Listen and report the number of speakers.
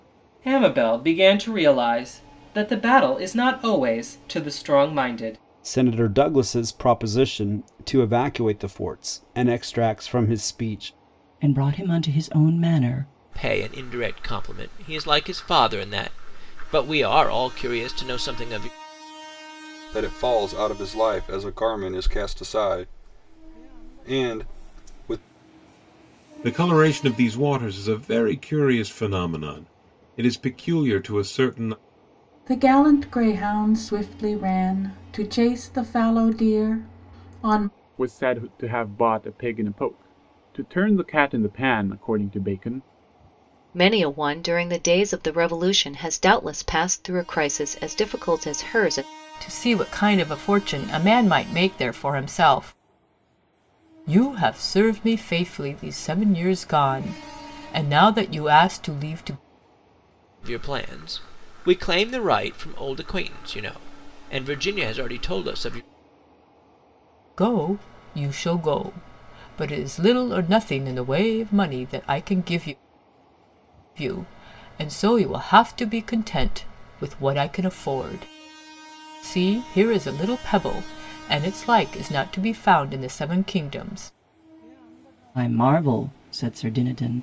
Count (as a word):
ten